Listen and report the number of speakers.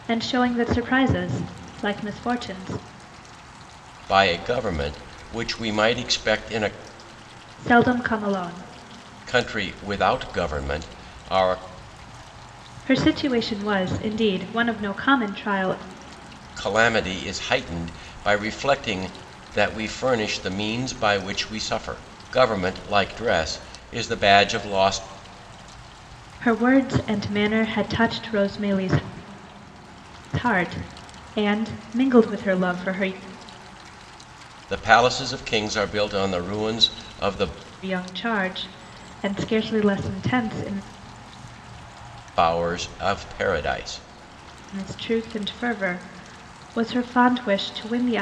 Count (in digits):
2